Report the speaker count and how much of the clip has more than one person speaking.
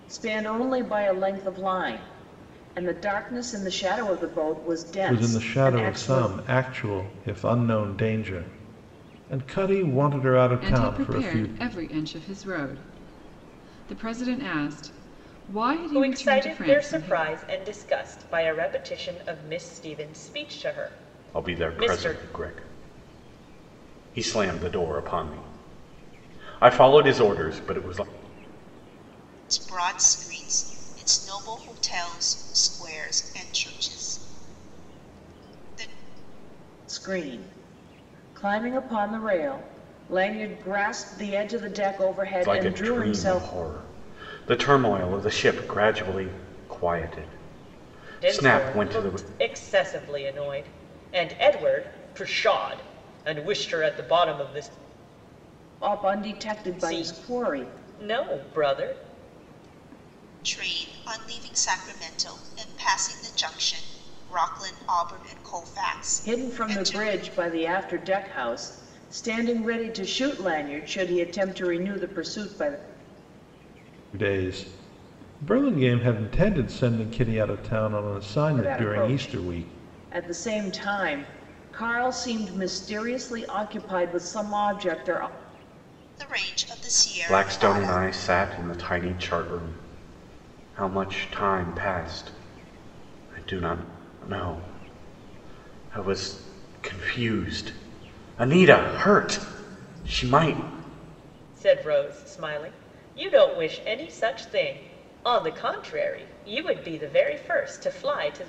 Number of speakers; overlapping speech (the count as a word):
six, about 10%